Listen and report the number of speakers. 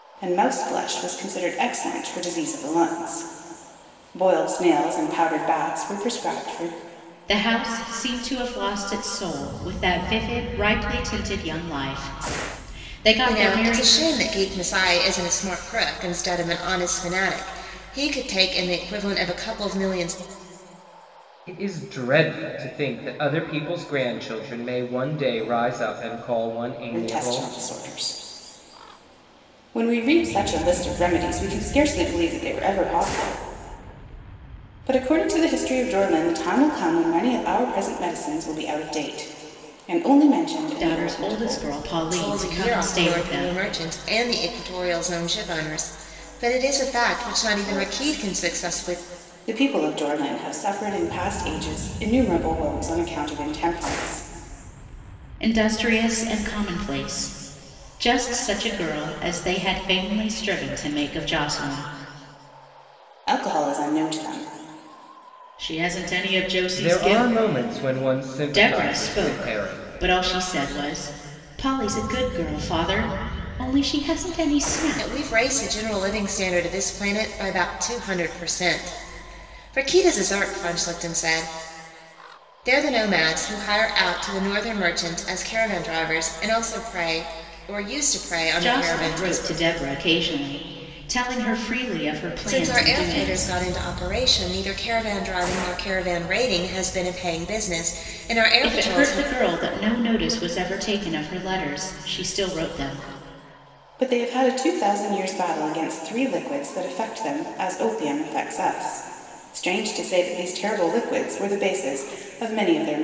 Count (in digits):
4